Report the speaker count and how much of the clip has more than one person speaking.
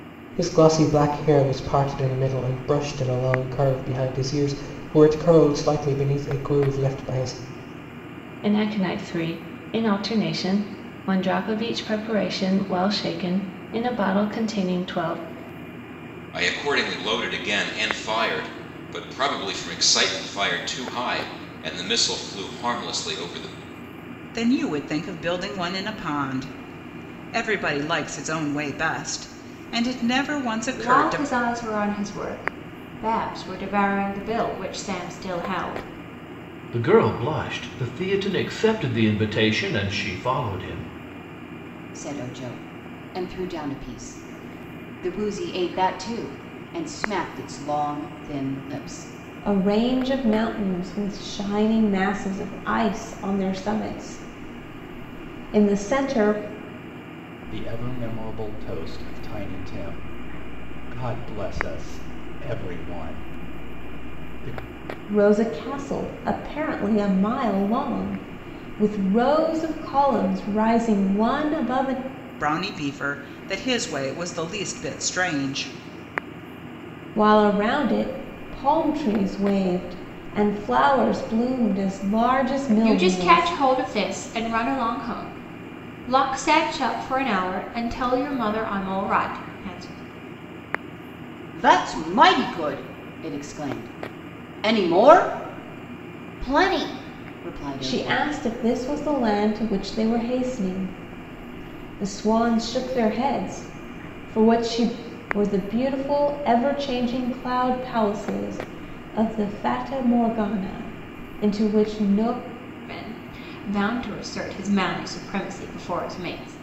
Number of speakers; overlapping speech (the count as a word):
nine, about 1%